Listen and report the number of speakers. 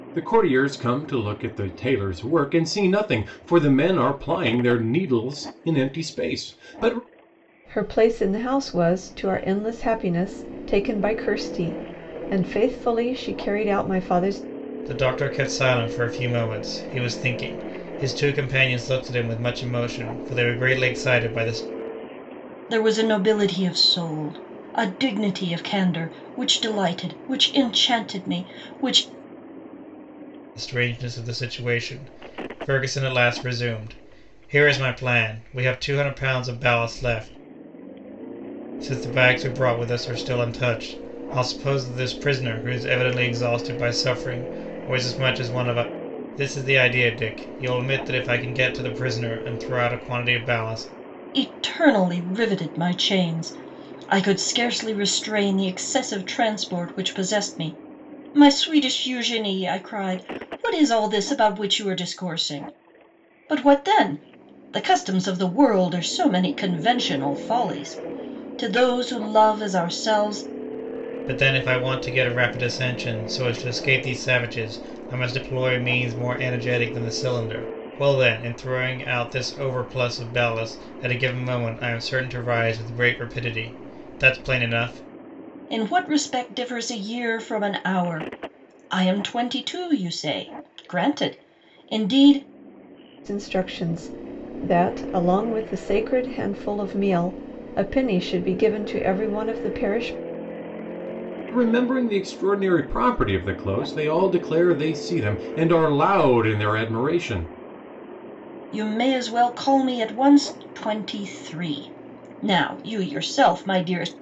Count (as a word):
four